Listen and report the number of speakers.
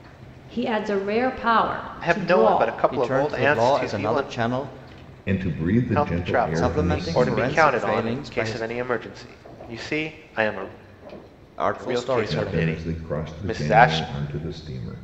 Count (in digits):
4